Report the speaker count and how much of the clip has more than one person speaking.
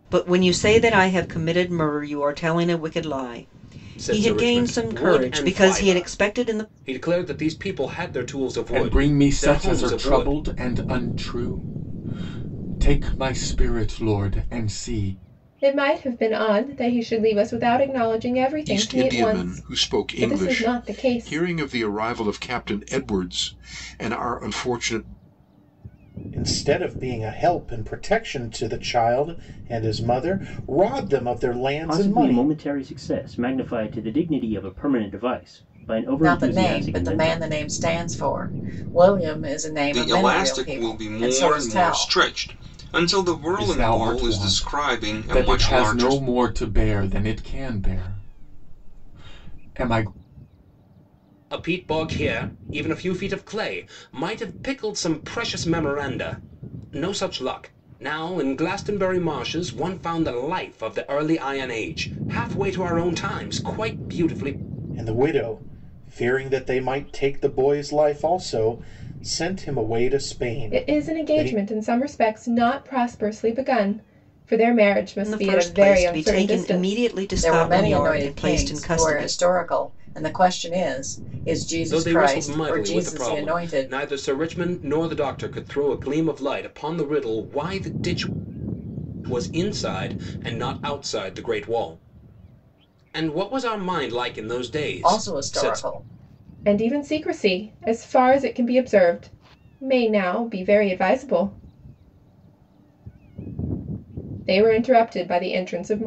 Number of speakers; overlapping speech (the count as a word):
nine, about 21%